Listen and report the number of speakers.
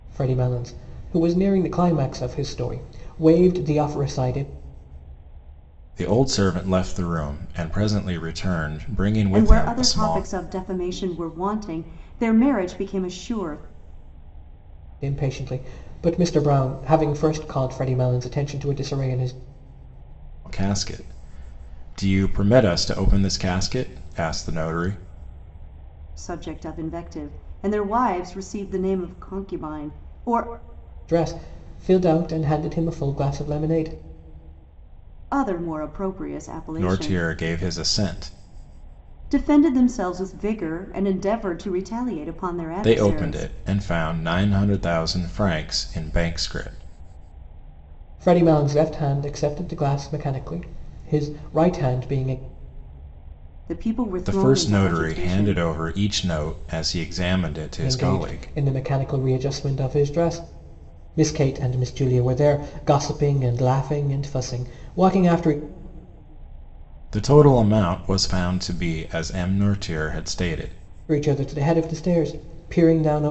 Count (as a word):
three